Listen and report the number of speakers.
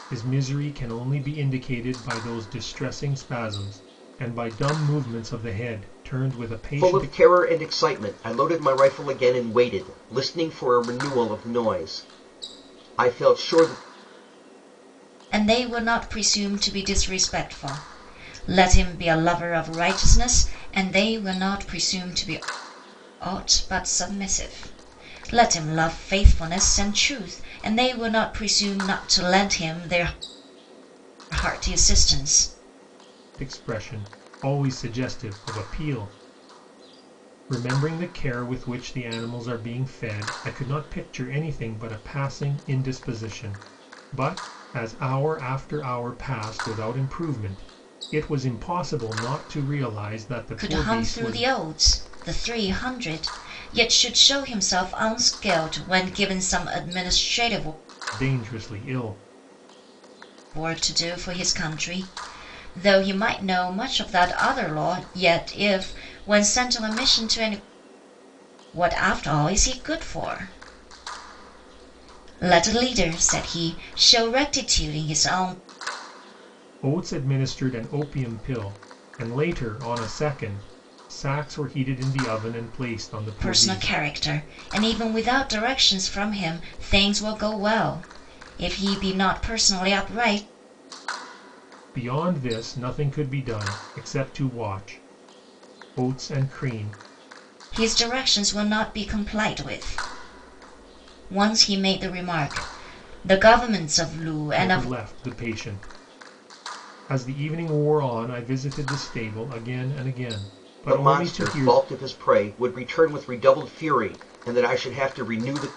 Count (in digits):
3